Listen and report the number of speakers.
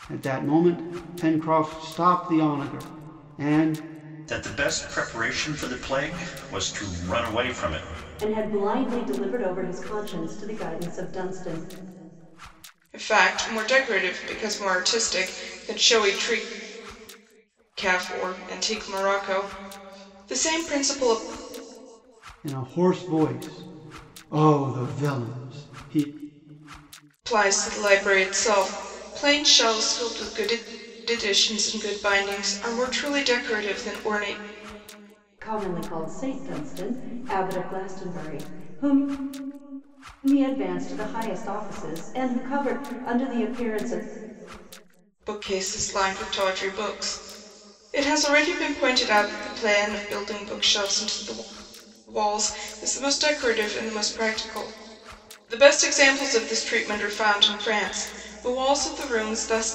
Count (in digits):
4